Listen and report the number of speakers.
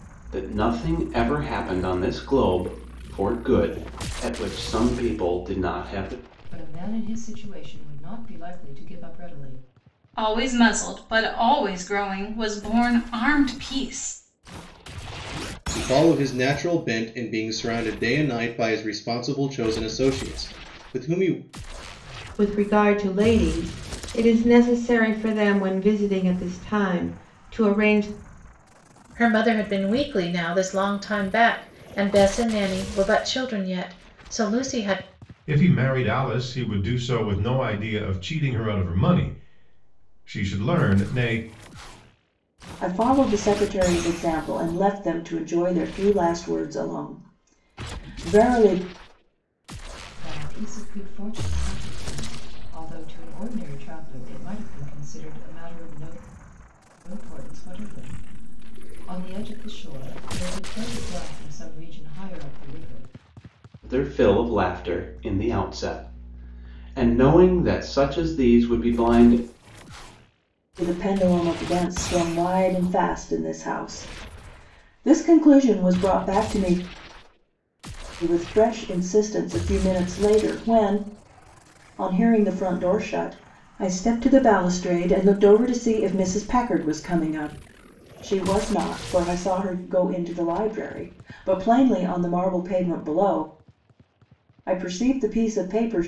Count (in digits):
8